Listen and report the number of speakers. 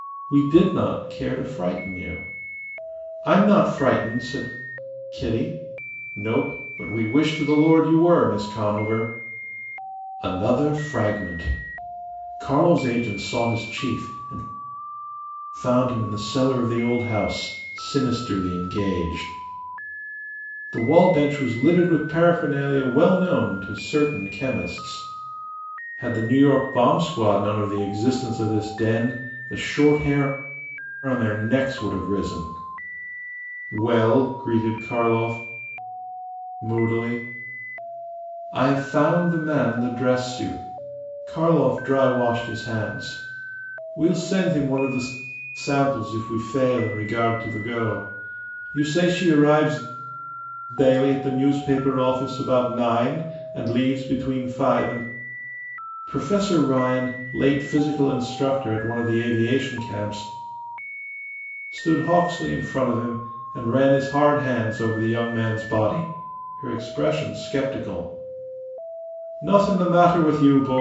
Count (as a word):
one